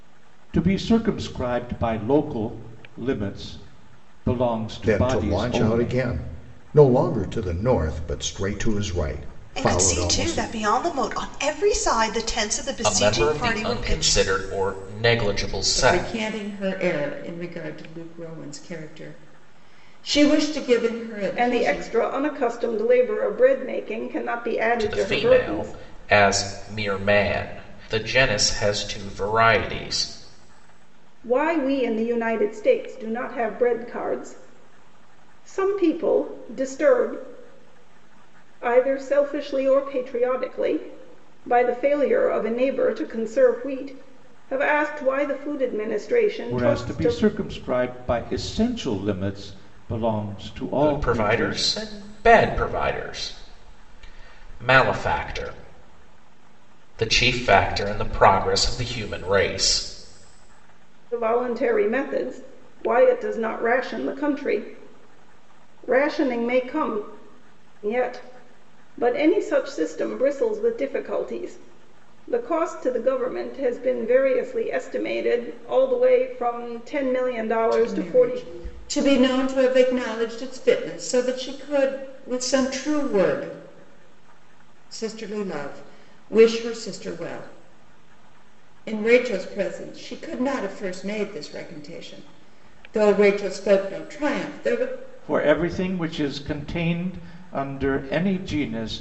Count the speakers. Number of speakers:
six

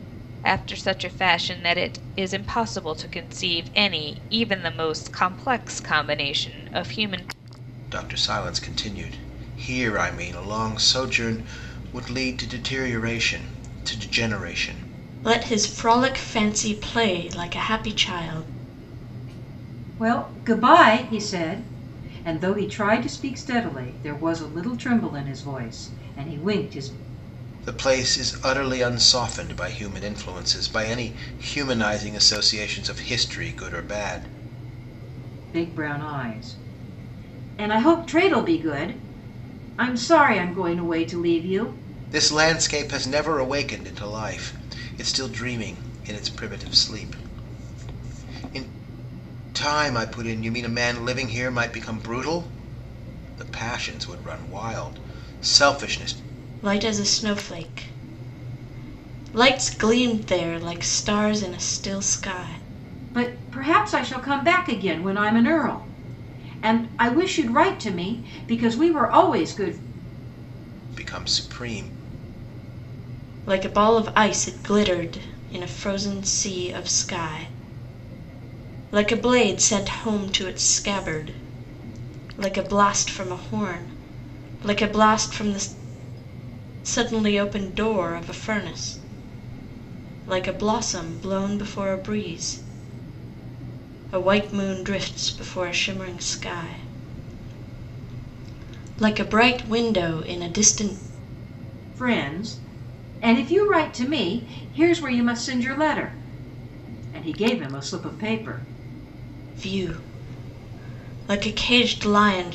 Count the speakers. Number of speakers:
four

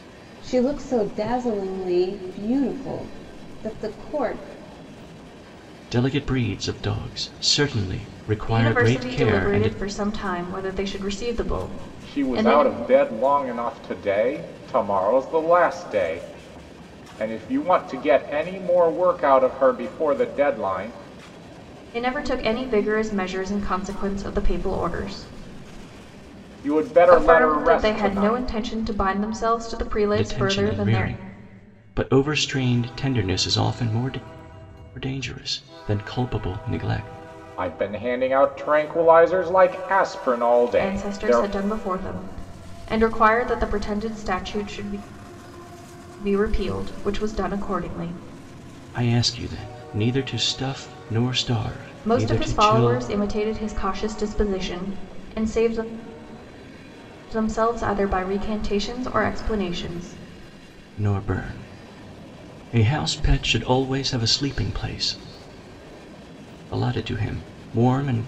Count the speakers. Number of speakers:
four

